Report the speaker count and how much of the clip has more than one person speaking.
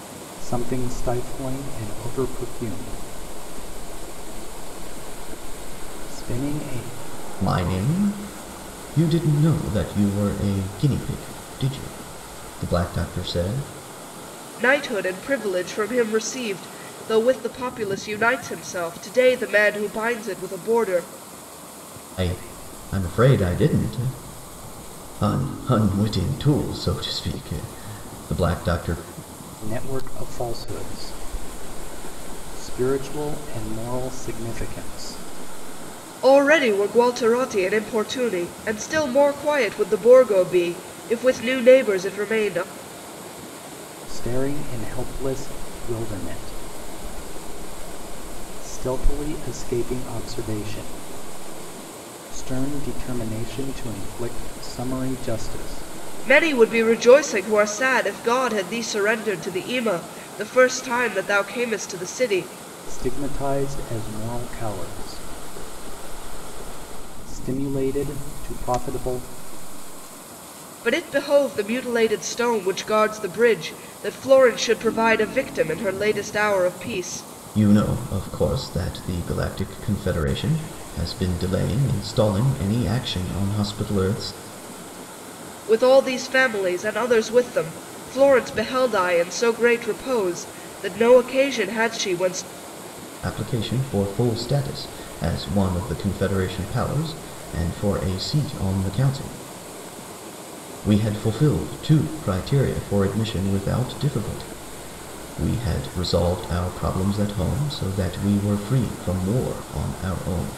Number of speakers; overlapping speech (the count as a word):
three, no overlap